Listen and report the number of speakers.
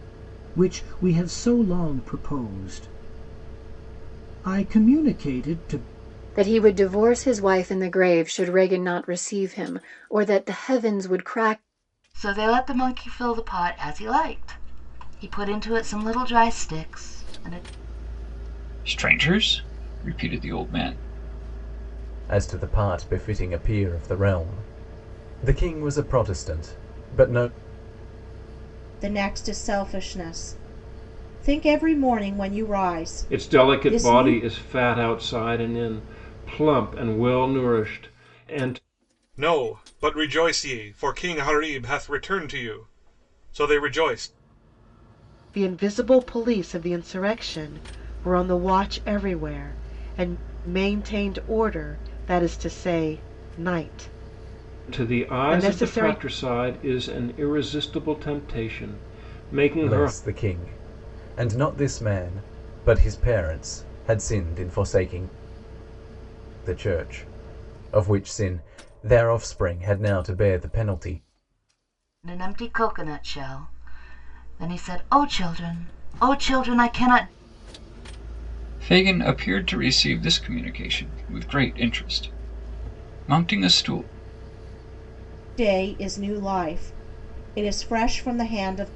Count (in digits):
9